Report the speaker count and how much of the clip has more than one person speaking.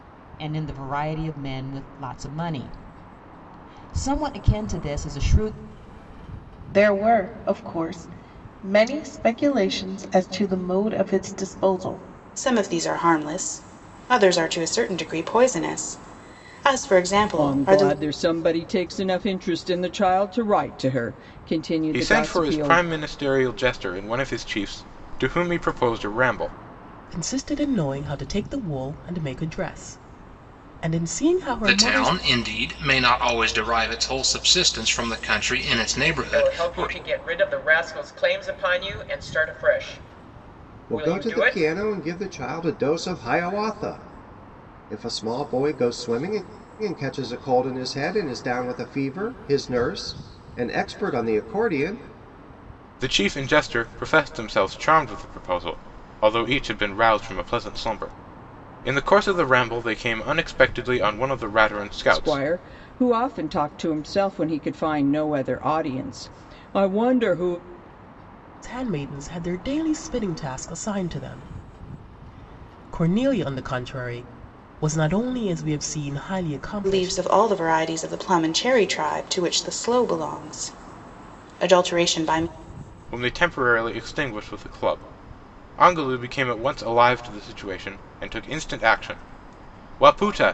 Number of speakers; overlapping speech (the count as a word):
nine, about 5%